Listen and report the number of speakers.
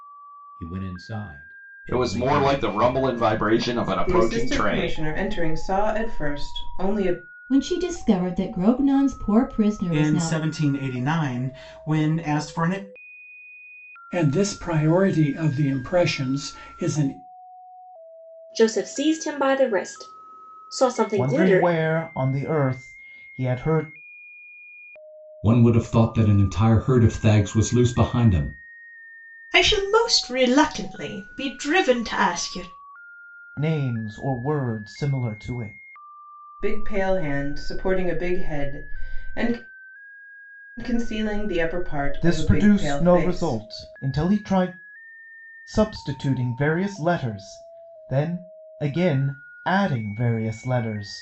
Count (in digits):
10